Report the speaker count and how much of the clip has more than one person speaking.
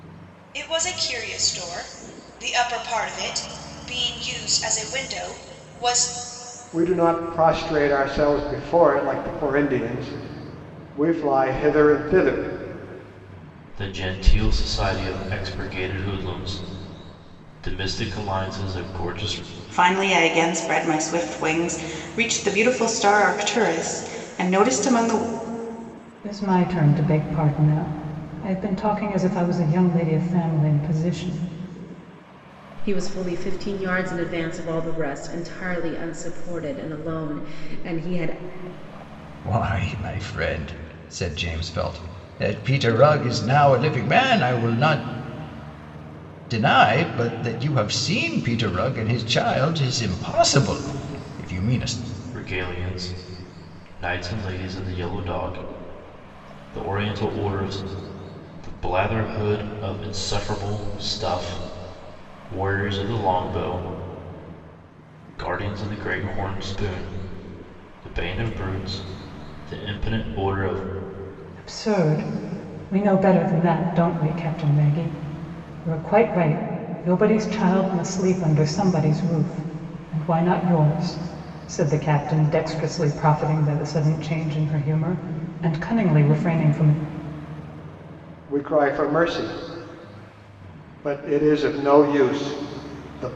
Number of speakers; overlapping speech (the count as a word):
seven, no overlap